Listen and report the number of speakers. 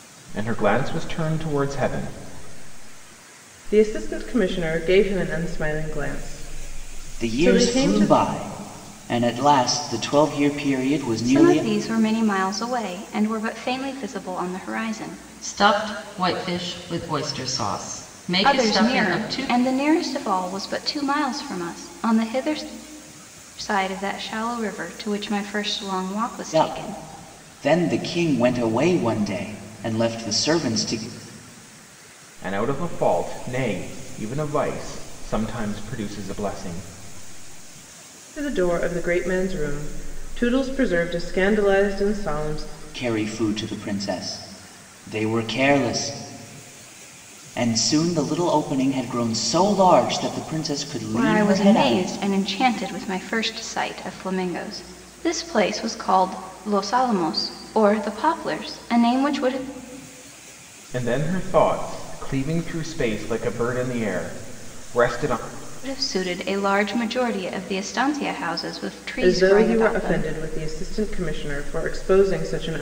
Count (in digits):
5